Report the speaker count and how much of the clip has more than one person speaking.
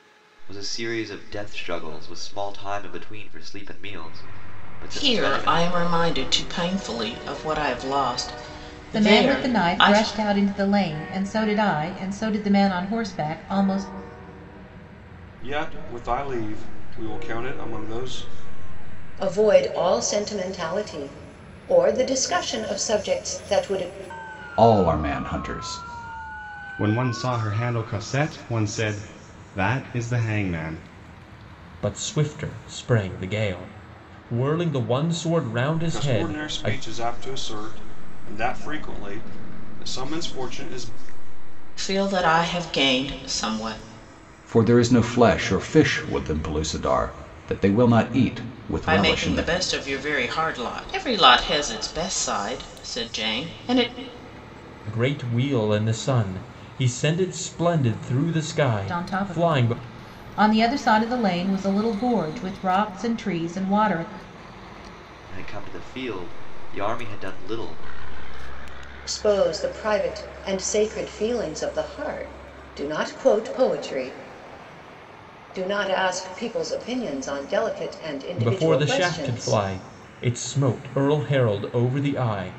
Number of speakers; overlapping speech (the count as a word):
eight, about 7%